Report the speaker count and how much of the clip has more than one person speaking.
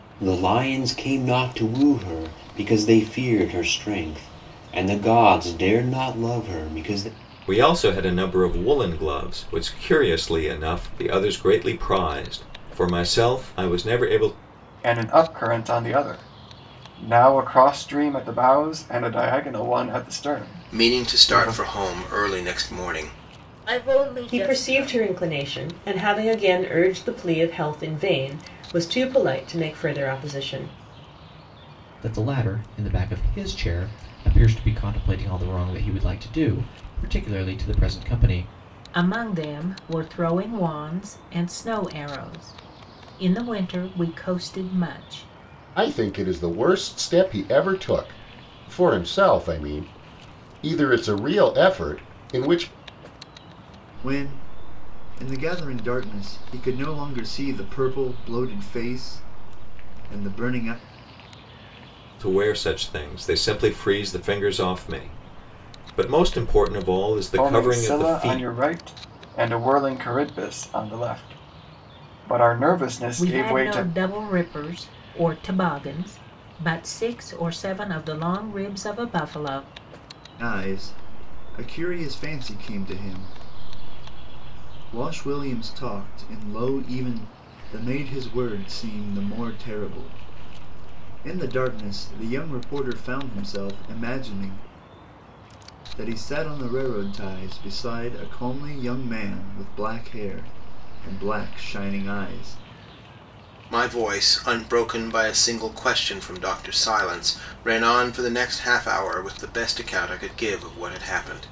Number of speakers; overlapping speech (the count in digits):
10, about 3%